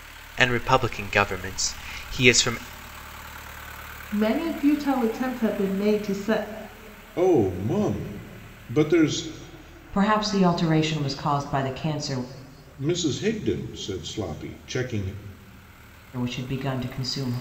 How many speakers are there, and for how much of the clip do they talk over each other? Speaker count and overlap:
4, no overlap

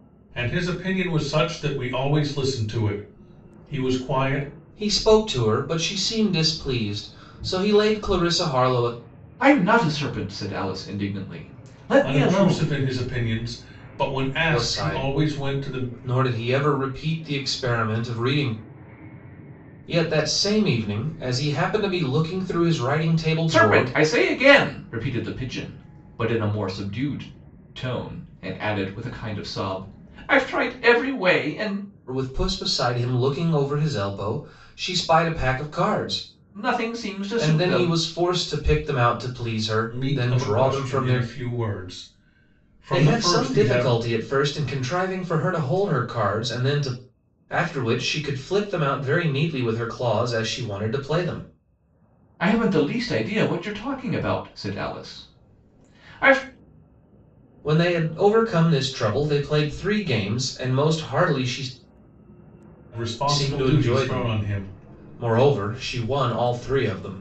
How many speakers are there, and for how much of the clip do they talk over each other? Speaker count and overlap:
3, about 10%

